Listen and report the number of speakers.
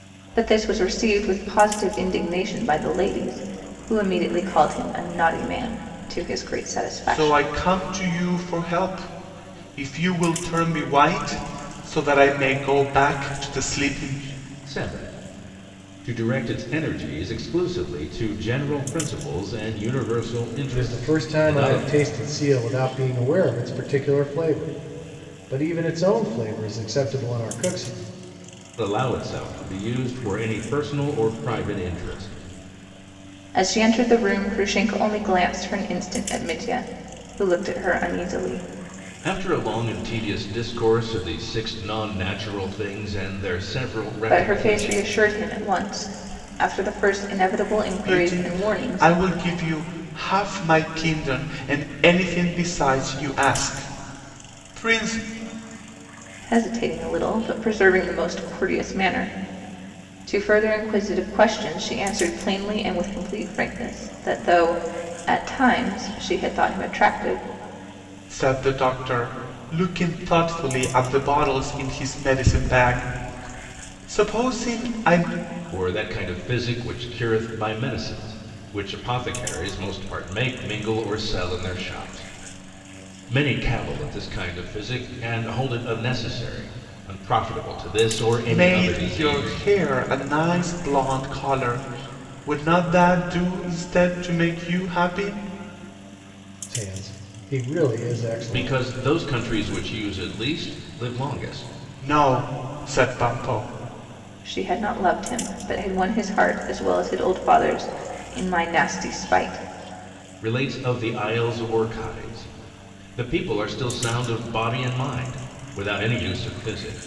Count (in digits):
4